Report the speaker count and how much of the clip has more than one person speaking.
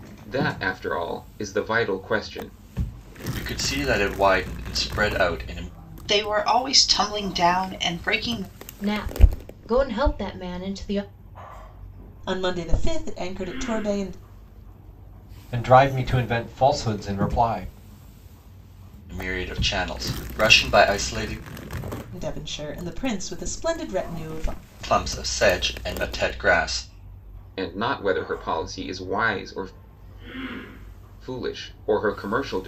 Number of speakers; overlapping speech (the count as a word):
six, no overlap